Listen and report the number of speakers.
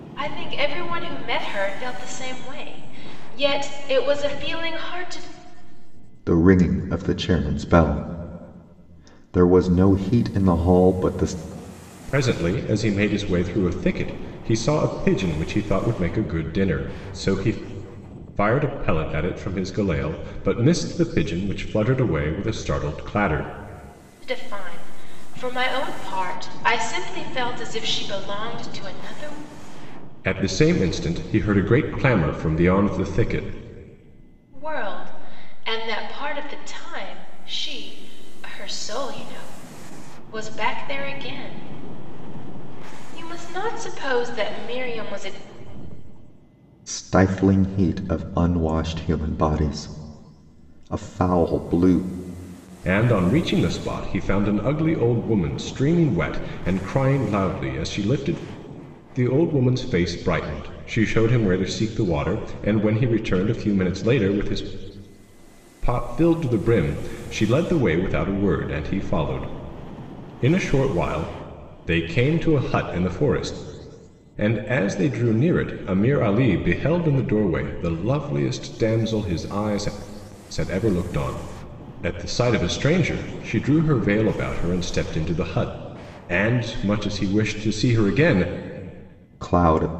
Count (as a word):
three